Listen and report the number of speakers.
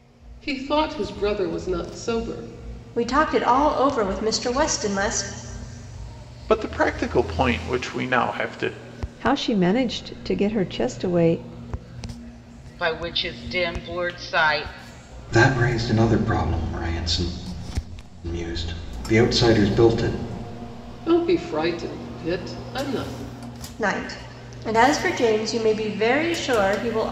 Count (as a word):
six